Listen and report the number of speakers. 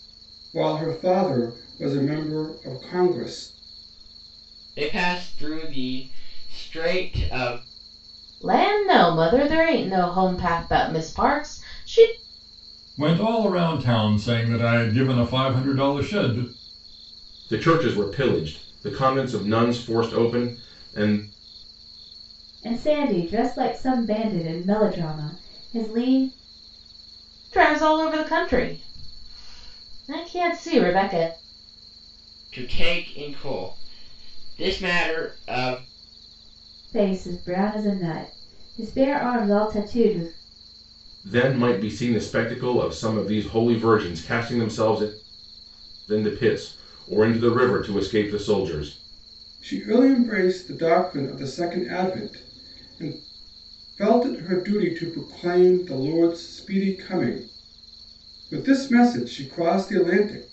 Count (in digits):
6